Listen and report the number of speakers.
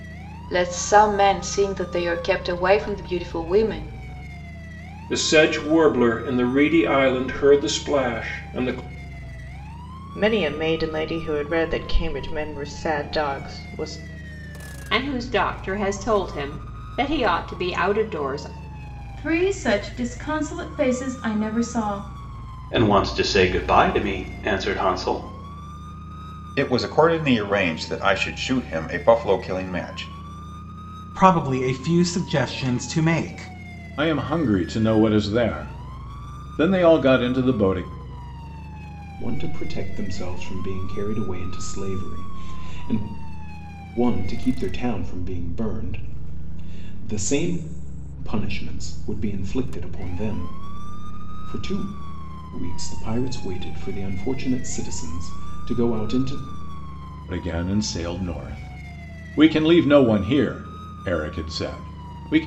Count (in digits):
10